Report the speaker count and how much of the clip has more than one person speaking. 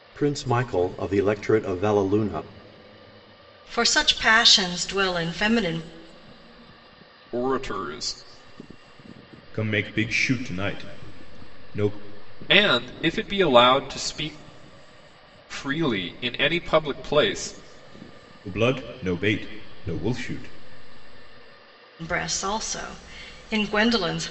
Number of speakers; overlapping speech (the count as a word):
four, no overlap